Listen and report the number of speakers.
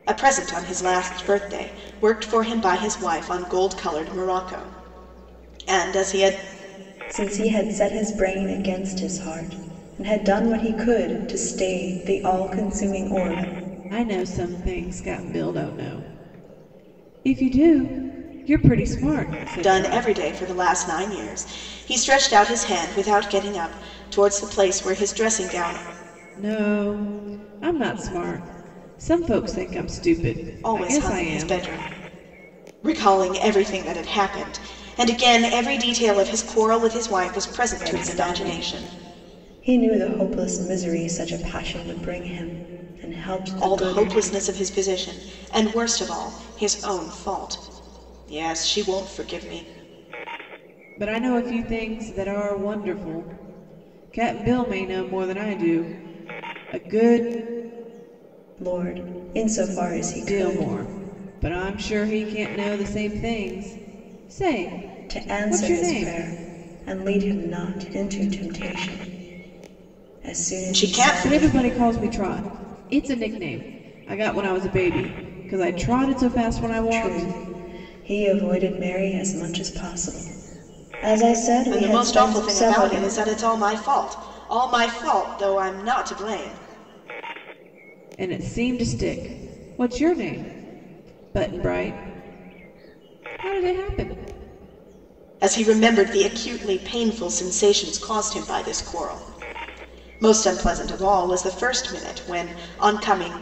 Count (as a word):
three